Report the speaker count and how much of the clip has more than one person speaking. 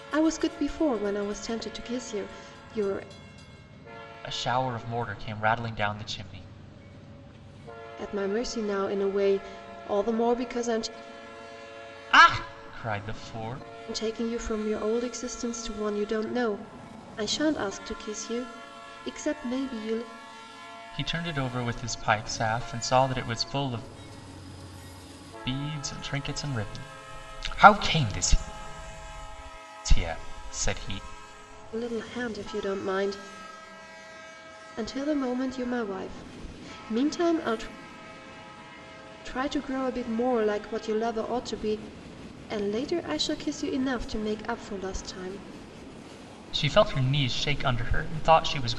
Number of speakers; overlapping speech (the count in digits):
2, no overlap